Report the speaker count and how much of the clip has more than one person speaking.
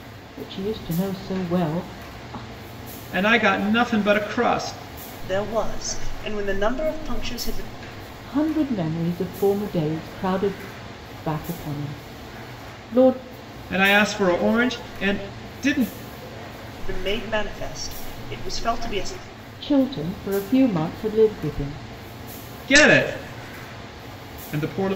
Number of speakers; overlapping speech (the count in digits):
3, no overlap